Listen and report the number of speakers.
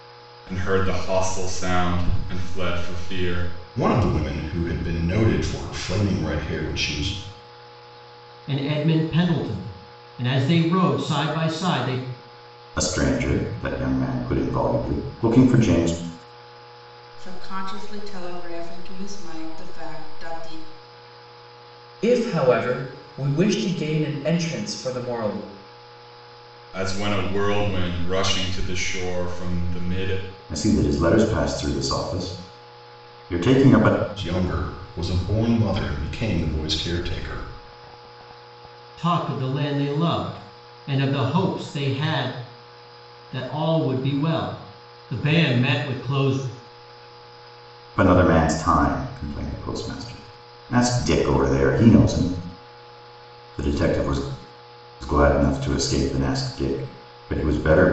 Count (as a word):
six